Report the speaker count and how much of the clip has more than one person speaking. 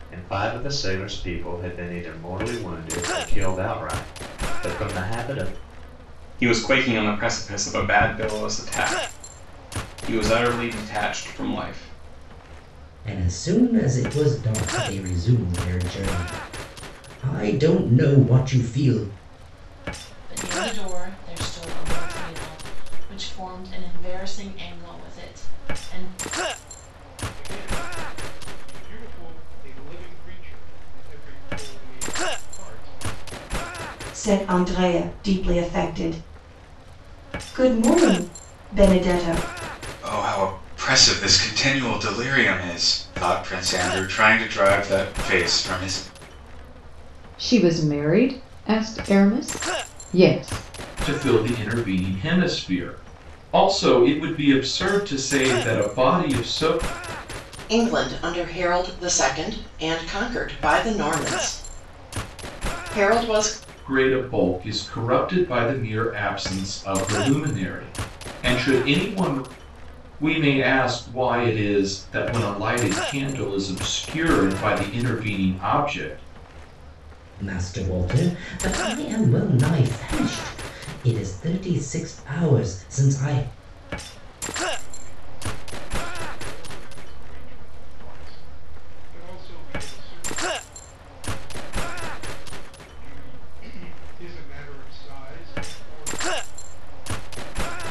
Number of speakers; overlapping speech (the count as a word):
ten, no overlap